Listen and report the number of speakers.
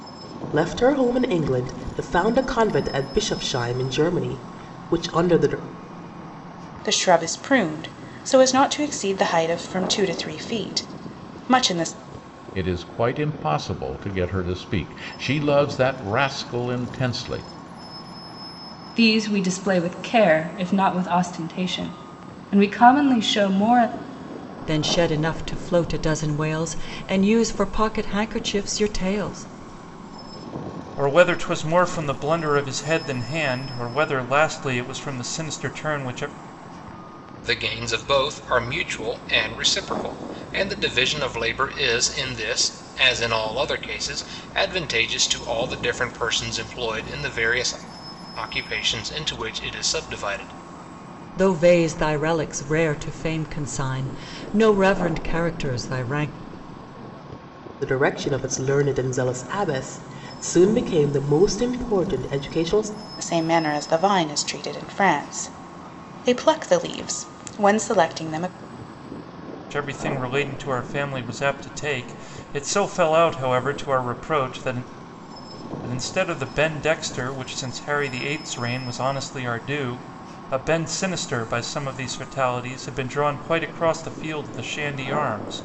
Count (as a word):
seven